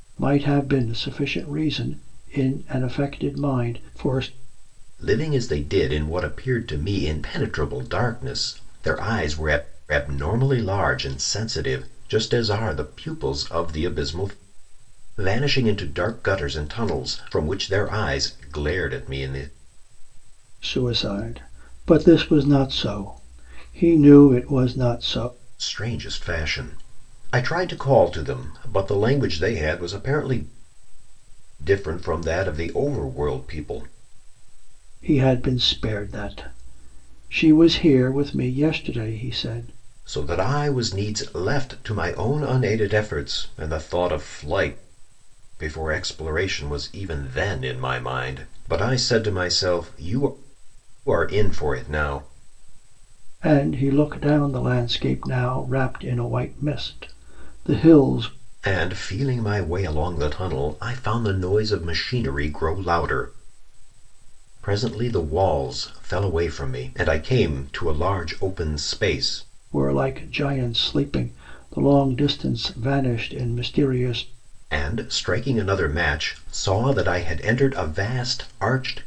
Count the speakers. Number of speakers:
two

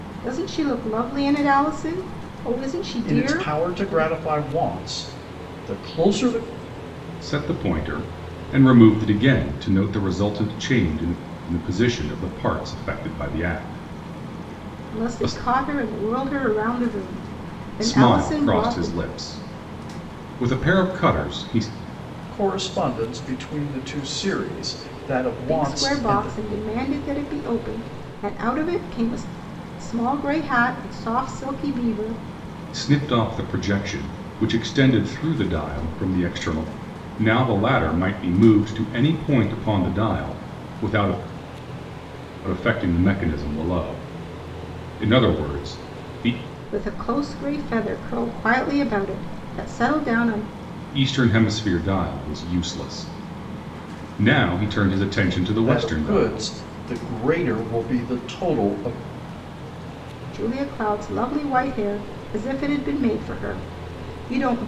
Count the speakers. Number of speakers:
three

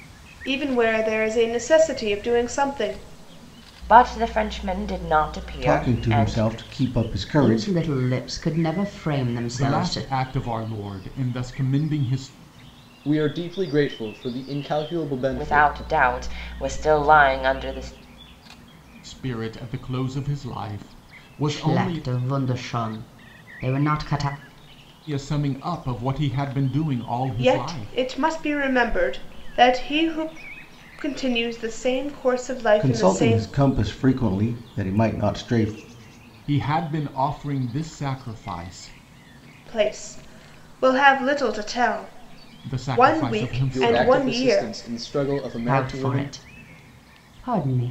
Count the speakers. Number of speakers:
six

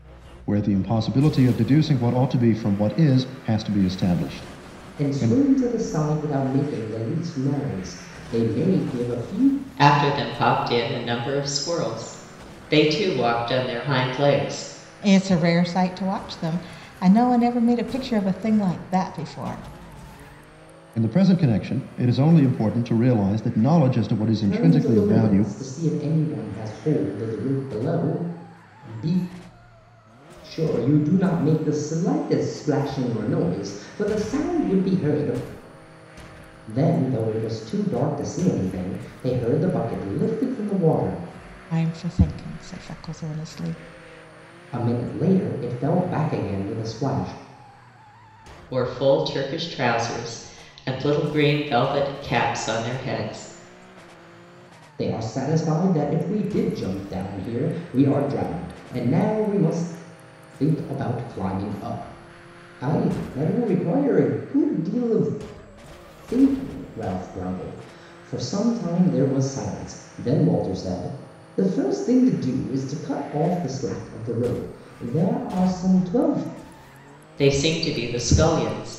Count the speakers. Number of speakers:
four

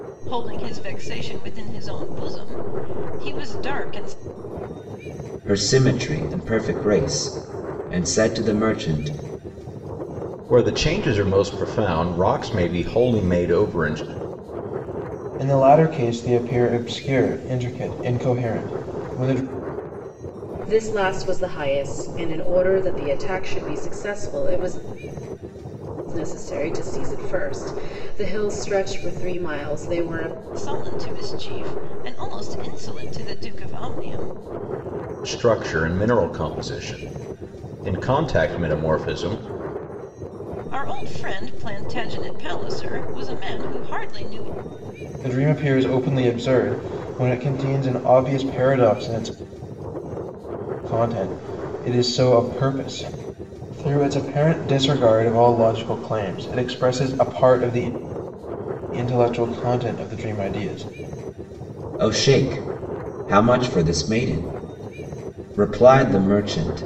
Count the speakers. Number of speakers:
five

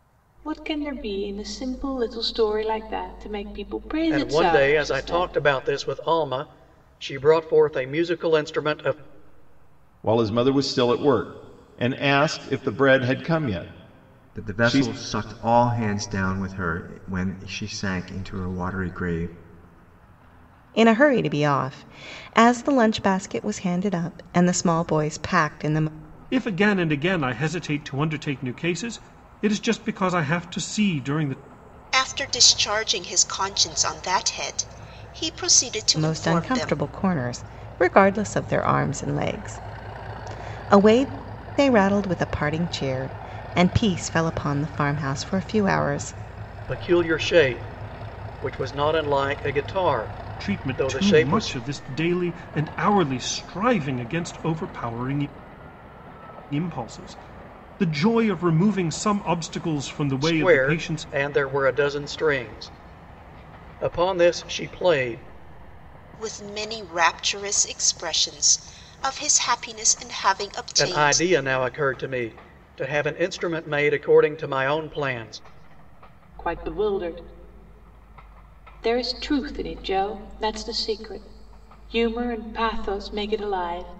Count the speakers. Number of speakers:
seven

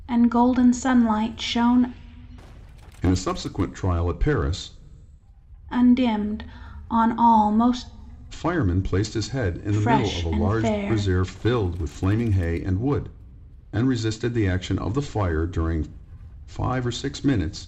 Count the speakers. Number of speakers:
two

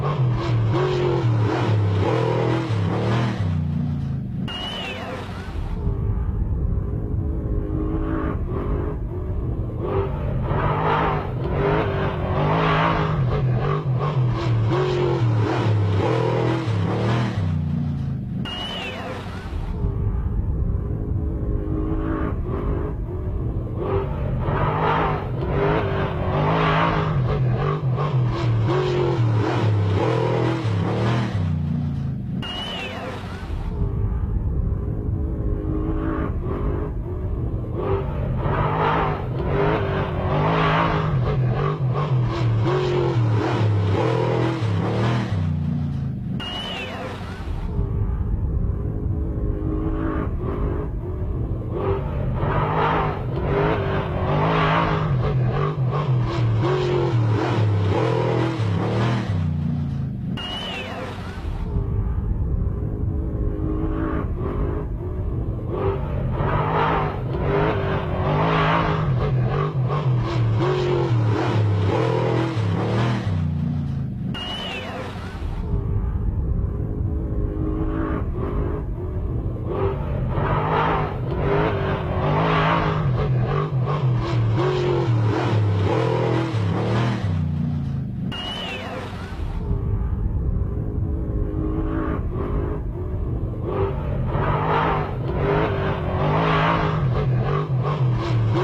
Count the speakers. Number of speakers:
zero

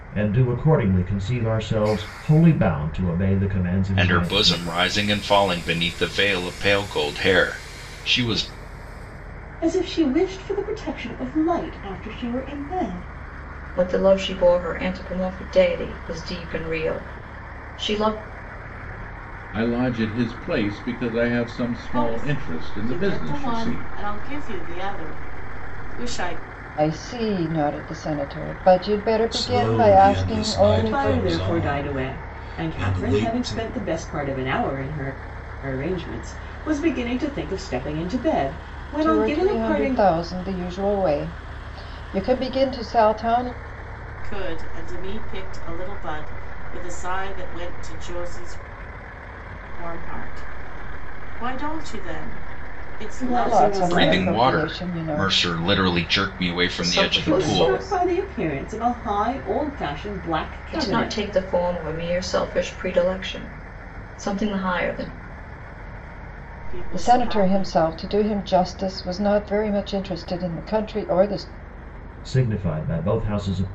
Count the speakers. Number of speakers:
eight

